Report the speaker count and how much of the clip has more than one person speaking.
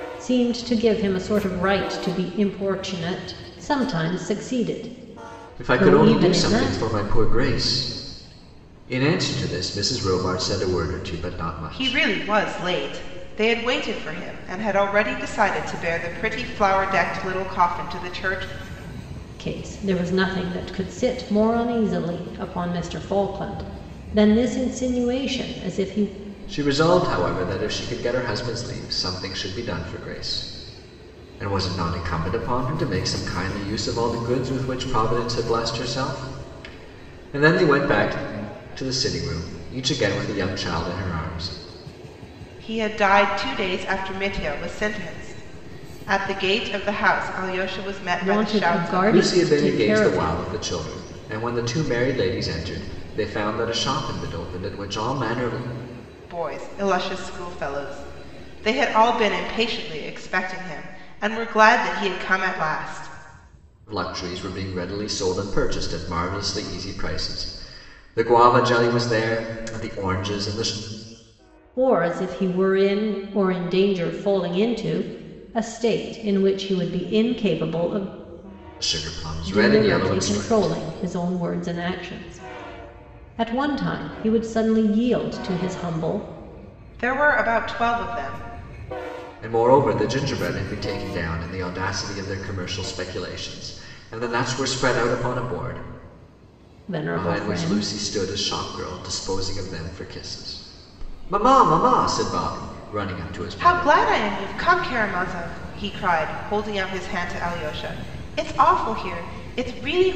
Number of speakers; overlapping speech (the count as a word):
three, about 6%